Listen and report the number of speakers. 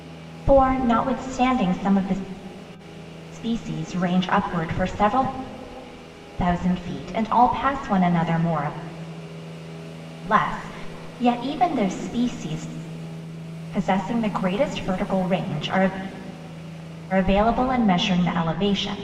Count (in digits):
1